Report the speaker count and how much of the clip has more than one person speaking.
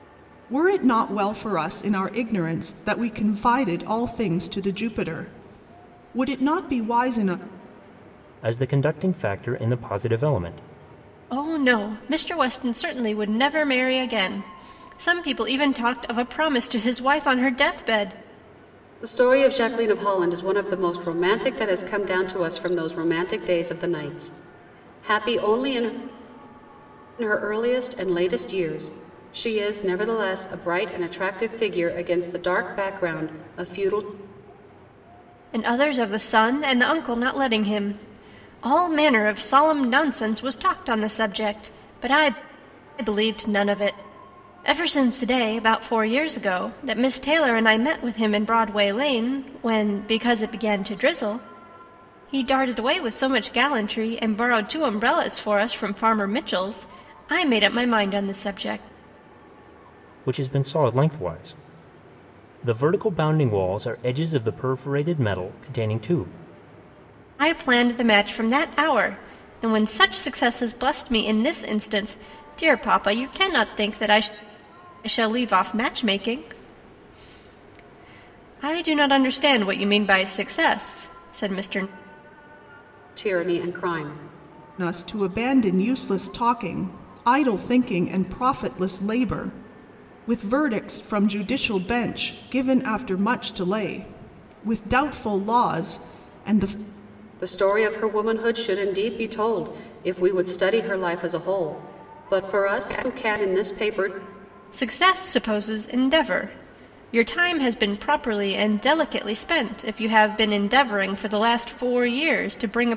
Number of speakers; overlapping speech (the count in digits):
4, no overlap